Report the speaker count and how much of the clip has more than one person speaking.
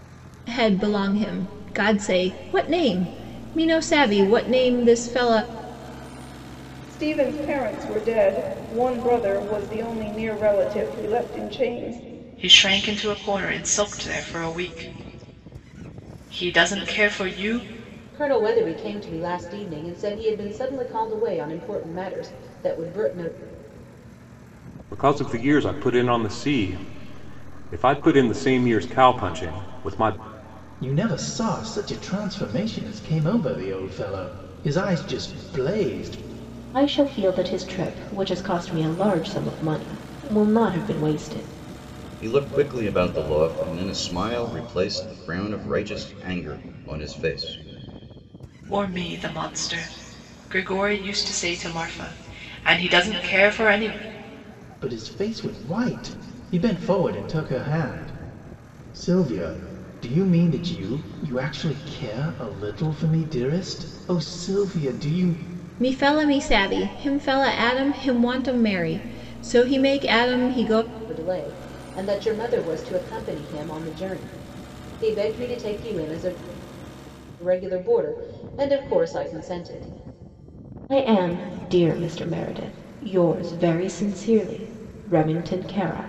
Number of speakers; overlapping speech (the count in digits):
8, no overlap